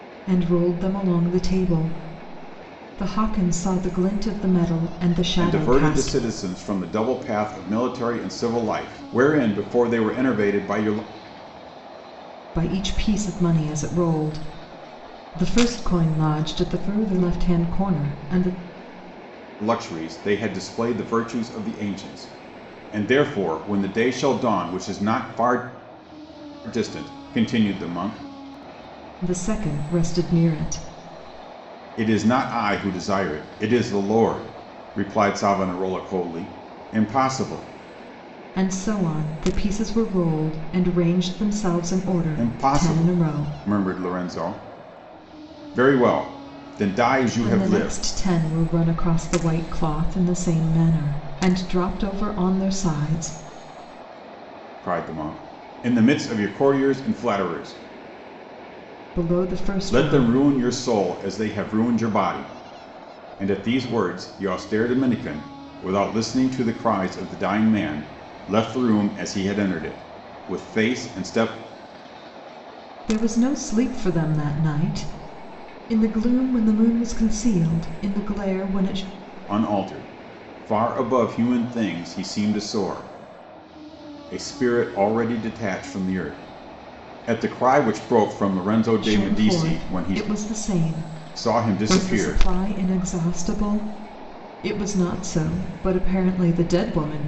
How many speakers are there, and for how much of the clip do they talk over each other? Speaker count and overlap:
two, about 5%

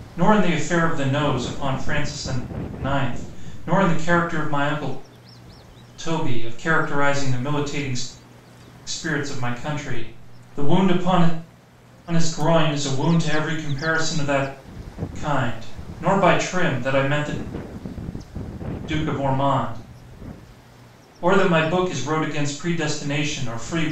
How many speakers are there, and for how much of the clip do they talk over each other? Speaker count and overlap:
one, no overlap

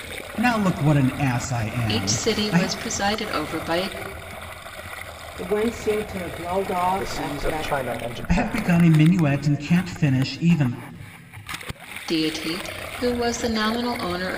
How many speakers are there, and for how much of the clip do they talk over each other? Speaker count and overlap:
four, about 15%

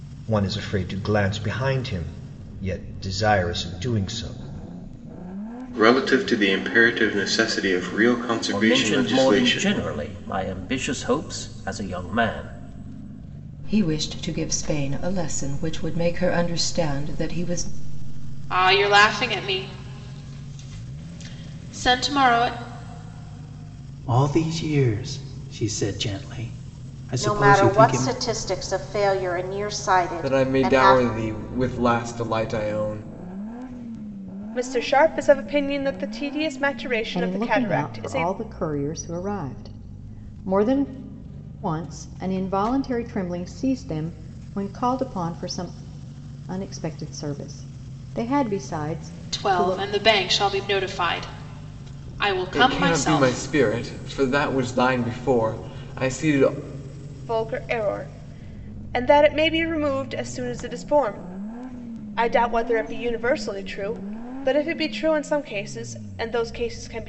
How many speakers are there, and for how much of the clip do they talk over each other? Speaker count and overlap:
ten, about 9%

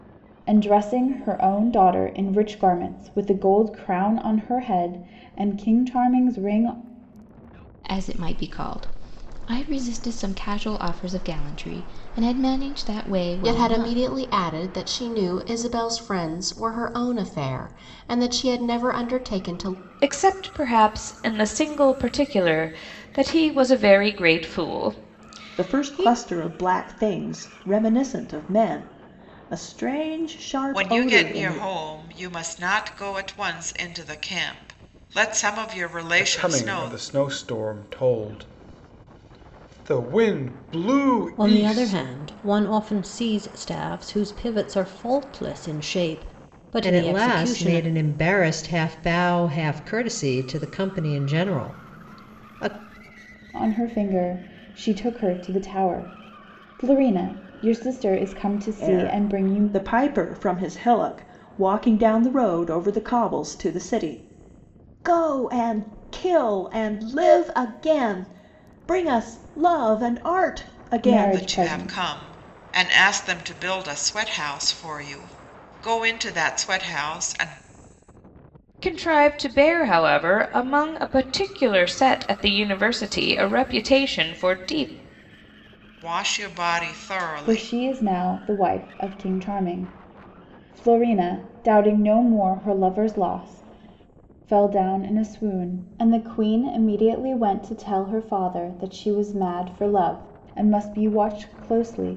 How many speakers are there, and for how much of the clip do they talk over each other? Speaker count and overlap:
nine, about 7%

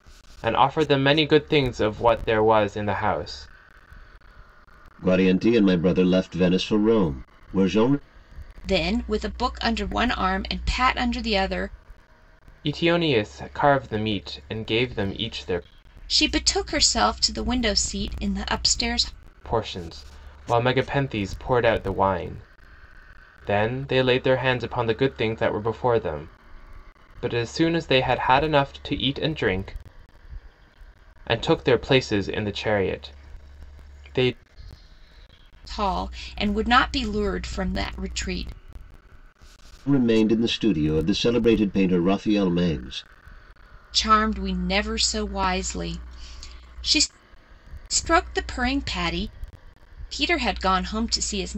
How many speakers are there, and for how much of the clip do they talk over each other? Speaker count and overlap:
three, no overlap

